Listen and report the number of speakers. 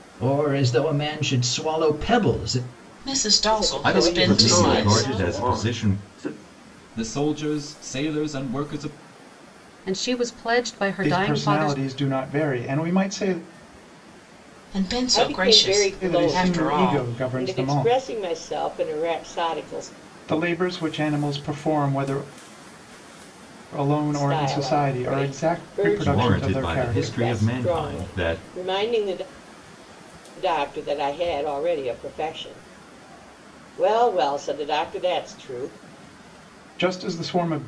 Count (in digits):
8